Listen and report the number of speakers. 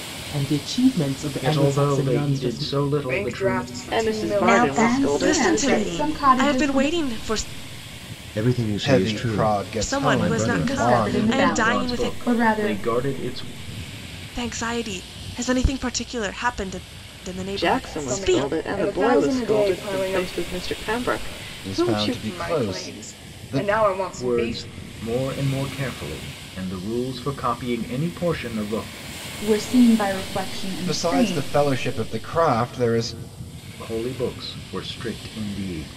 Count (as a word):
nine